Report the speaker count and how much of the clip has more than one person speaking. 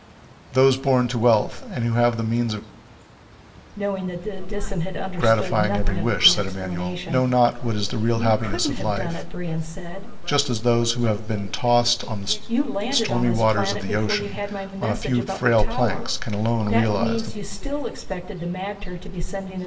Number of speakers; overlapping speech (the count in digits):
3, about 67%